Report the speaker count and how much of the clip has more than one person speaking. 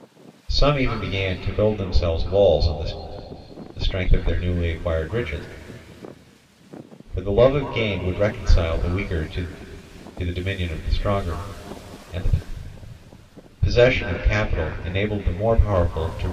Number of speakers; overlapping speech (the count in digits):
1, no overlap